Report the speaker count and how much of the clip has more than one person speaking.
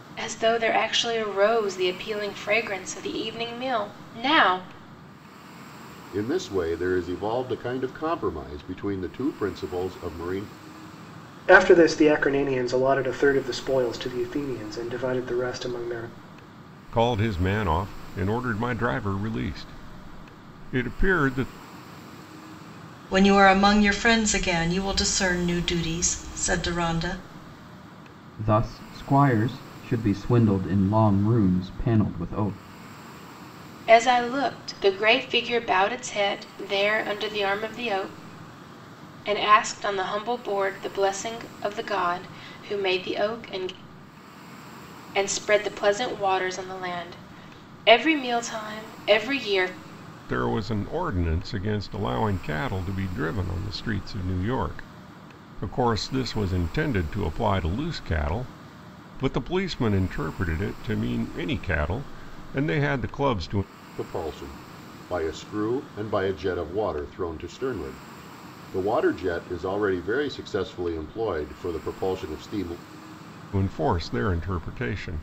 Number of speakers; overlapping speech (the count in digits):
6, no overlap